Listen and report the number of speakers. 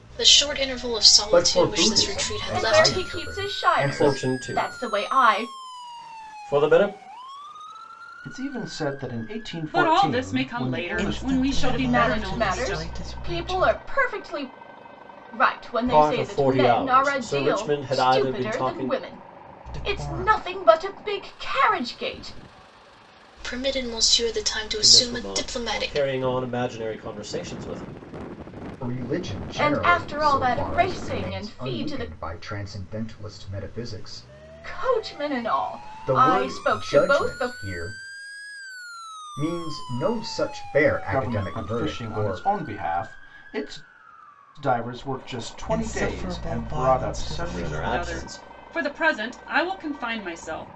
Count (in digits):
7